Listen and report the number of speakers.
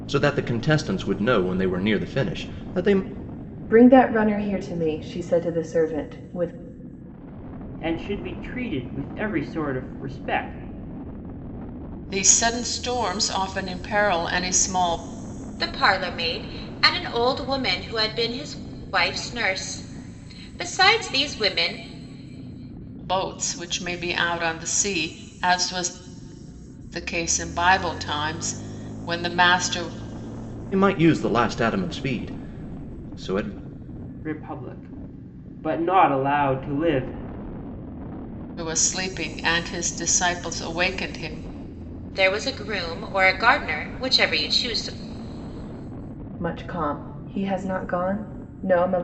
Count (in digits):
5